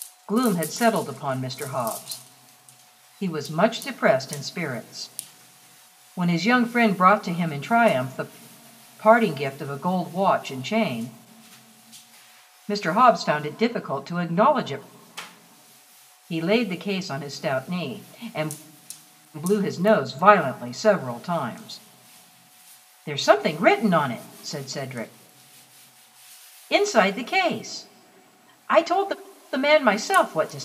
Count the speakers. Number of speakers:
1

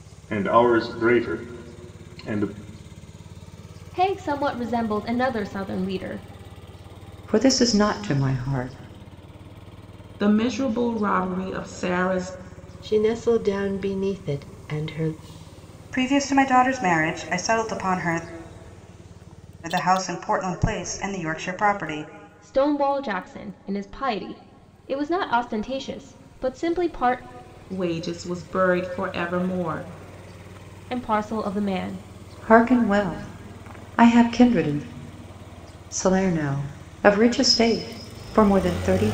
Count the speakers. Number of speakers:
6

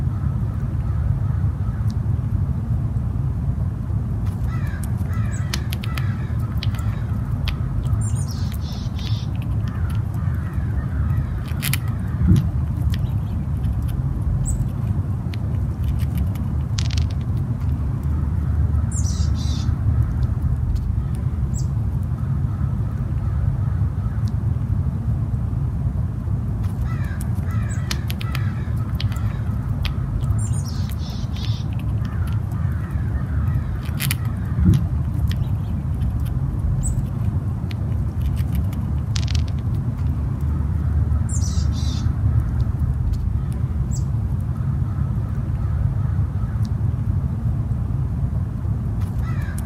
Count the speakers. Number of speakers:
0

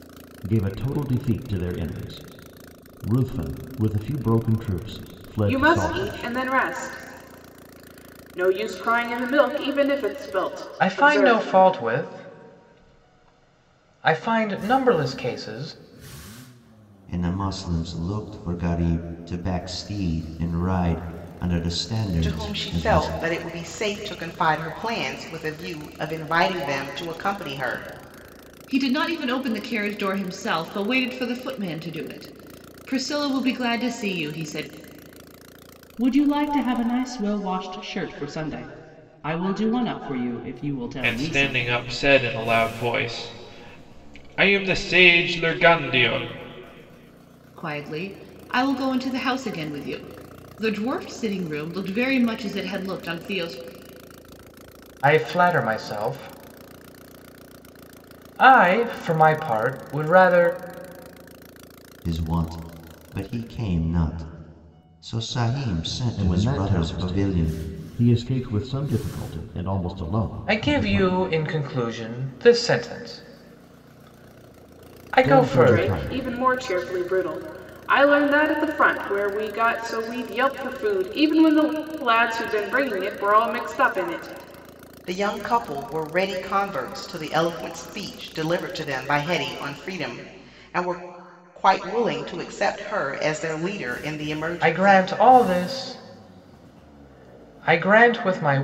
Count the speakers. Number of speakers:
8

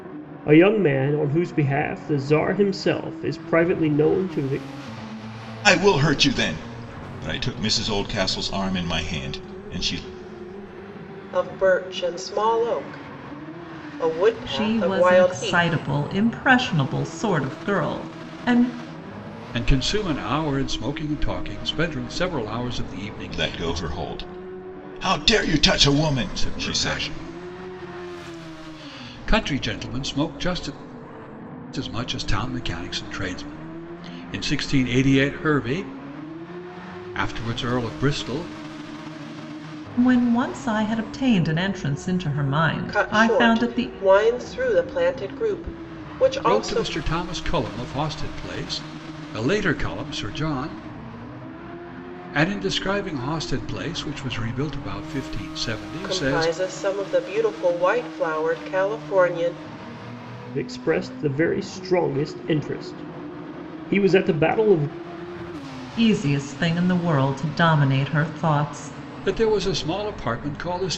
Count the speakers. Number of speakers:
5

